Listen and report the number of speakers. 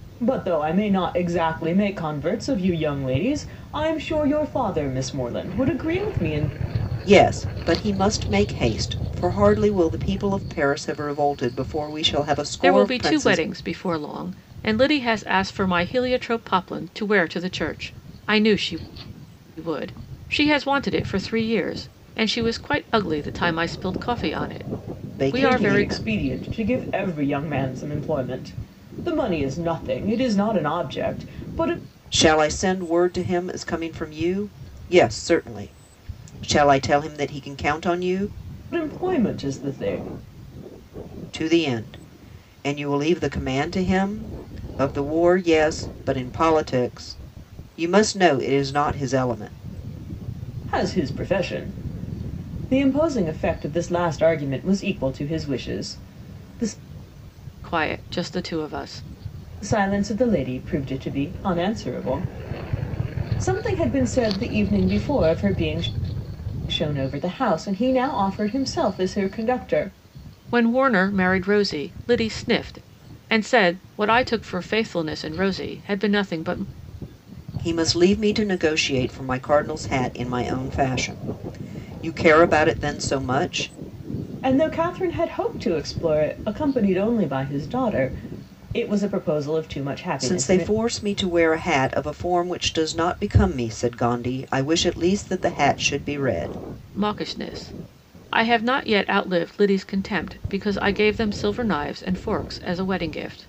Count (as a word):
three